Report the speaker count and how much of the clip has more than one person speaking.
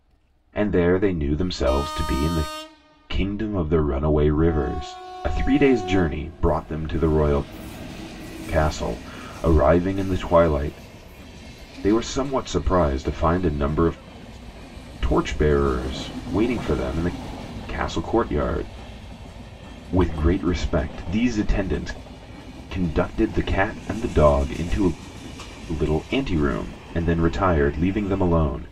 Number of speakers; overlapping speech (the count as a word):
one, no overlap